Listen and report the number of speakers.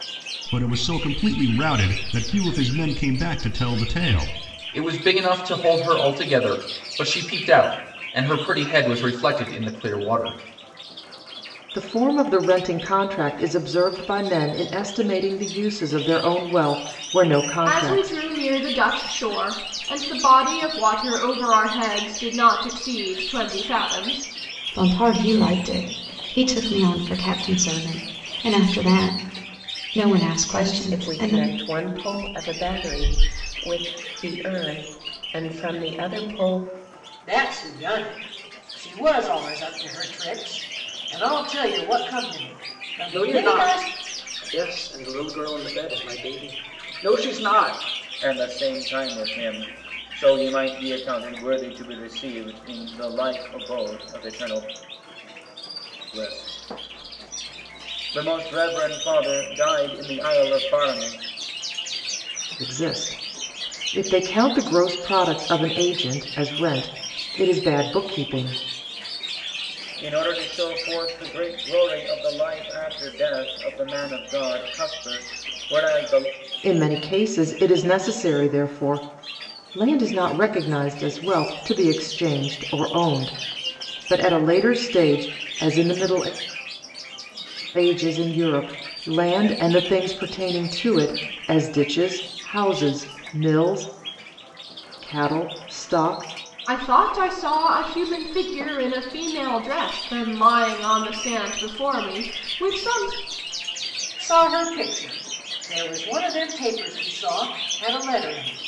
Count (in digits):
9